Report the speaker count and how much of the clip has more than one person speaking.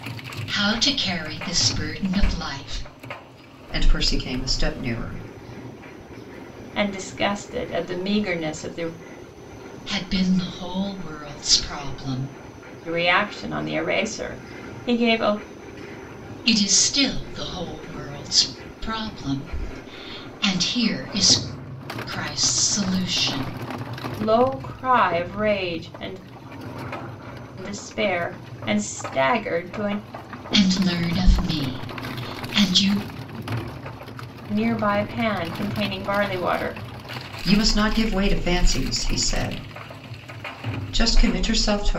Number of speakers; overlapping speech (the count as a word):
three, no overlap